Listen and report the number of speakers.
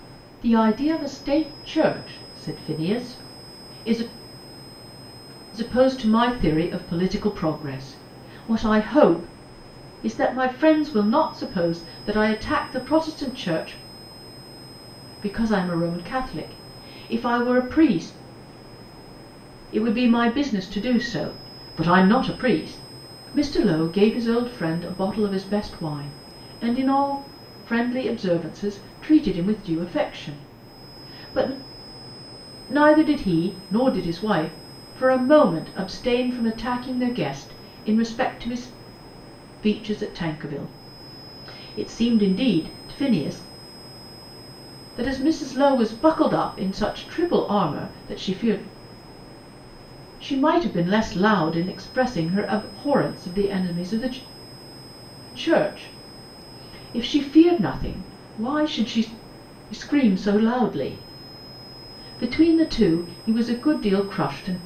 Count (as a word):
one